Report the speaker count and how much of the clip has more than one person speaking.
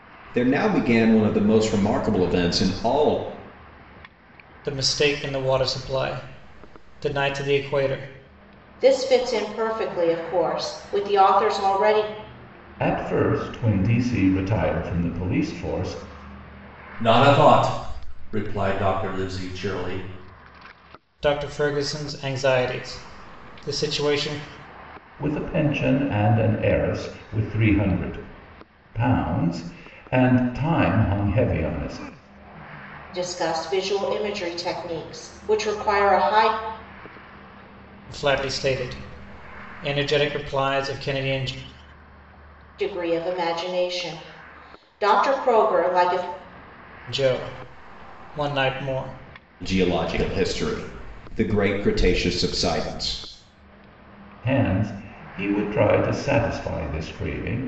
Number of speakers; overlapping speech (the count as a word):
five, no overlap